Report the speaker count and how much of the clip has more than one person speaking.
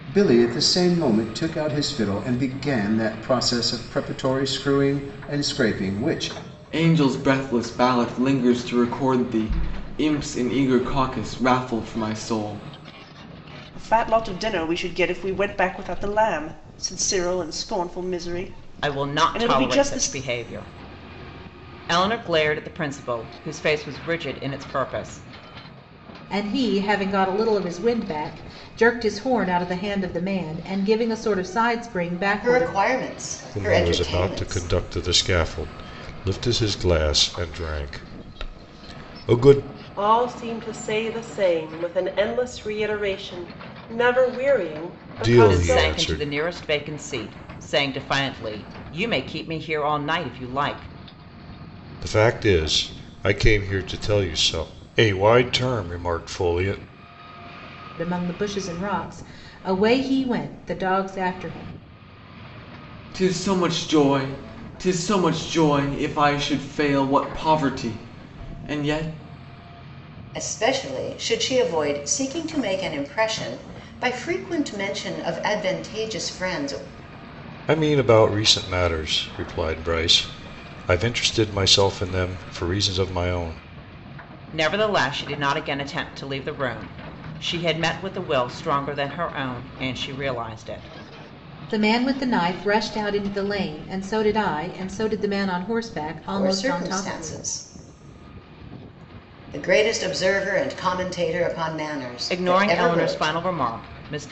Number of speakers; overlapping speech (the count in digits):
8, about 6%